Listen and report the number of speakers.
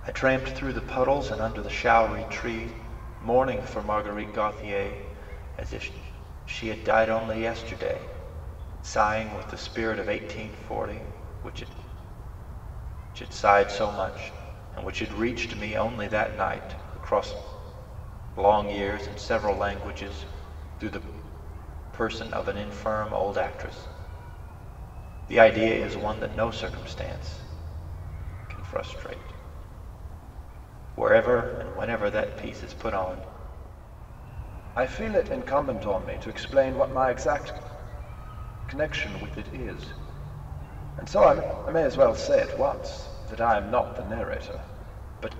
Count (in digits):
1